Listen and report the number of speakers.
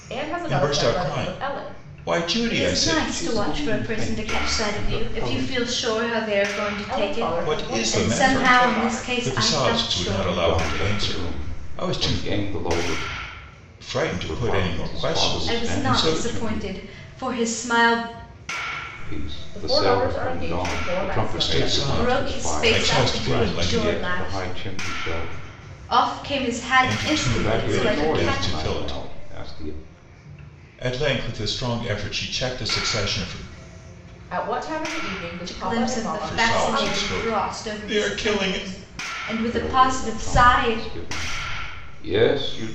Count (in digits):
4